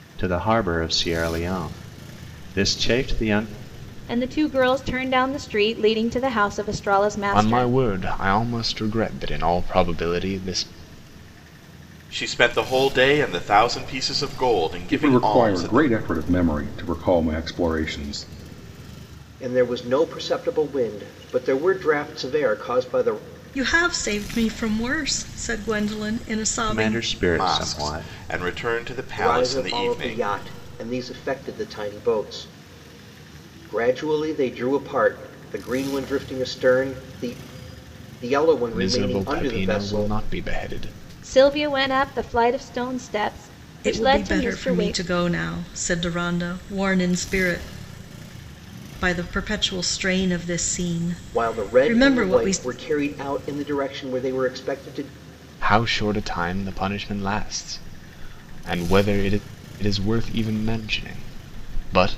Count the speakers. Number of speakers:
7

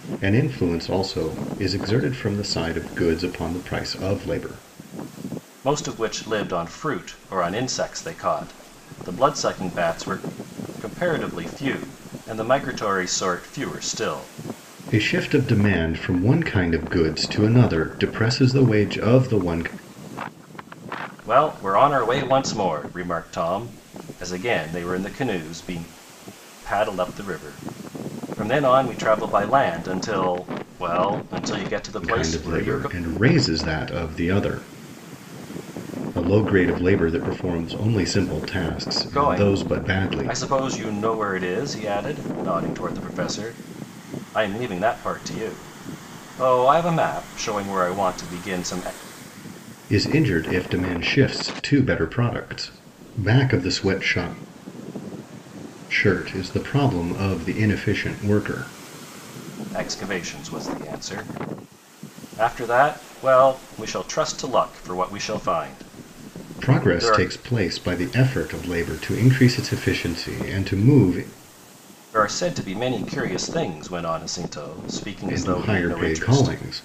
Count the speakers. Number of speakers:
2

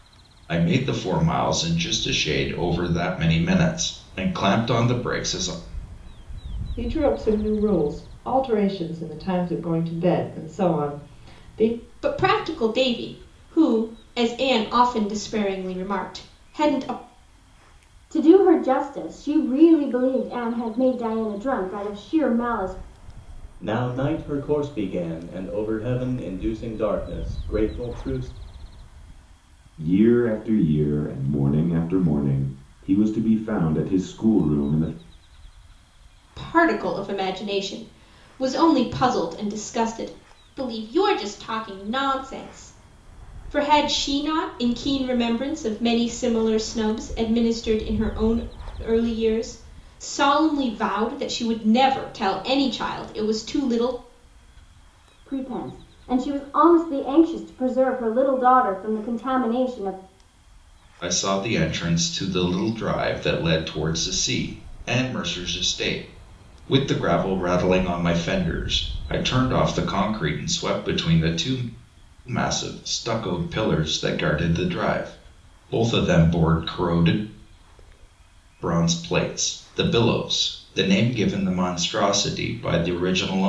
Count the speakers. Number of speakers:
6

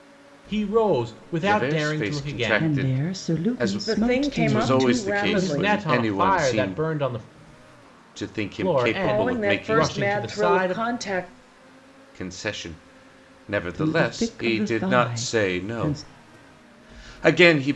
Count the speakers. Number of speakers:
4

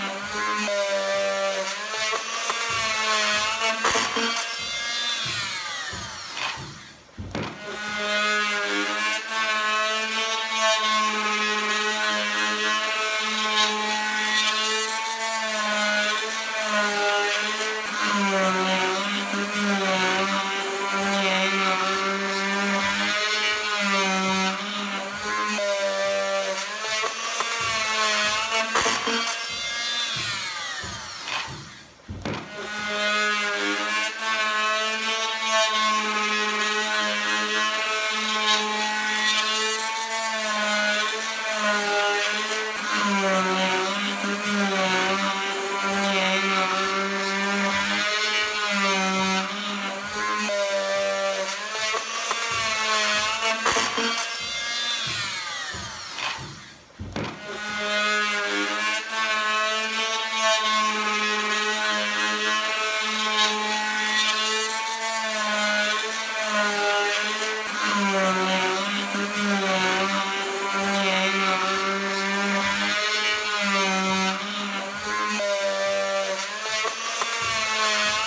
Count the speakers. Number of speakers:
0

